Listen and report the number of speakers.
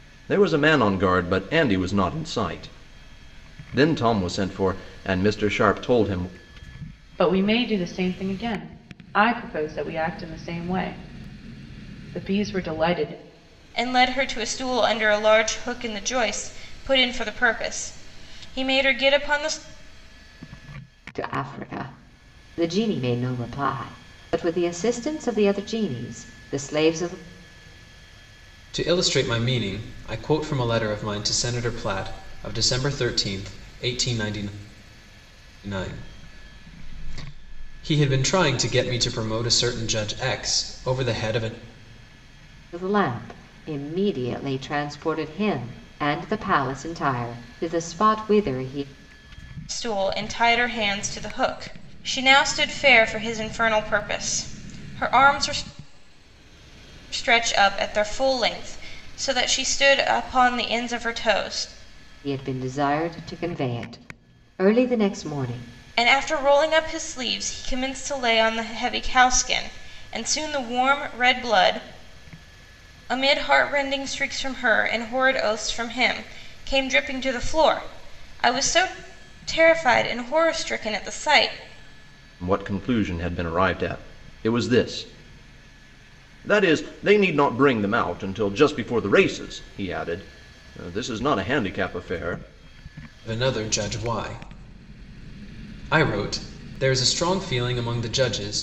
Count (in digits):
5